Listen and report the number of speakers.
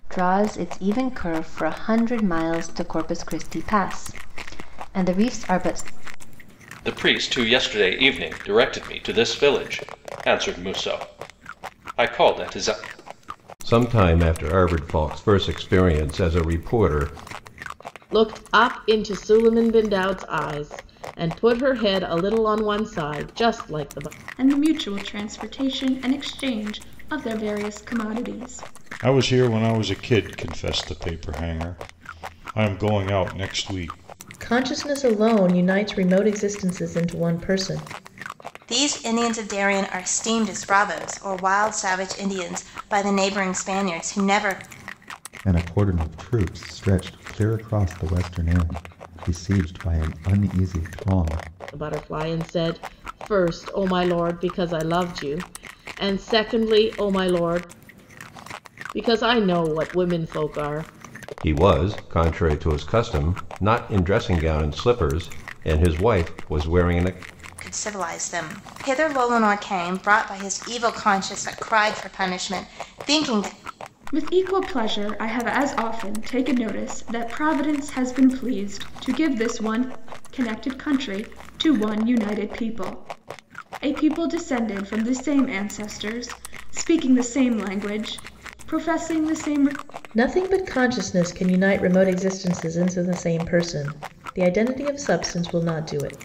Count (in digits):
9